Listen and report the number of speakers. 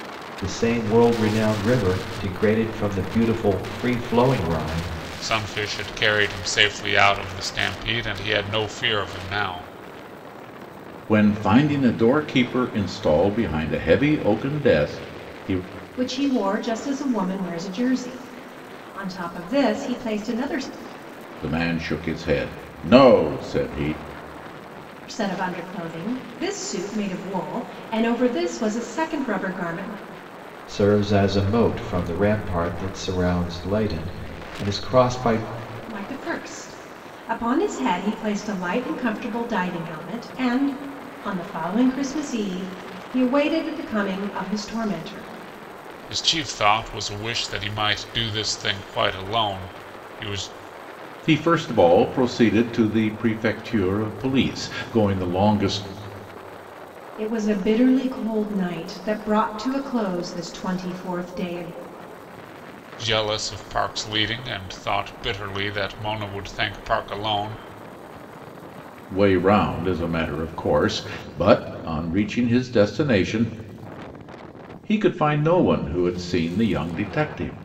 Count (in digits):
4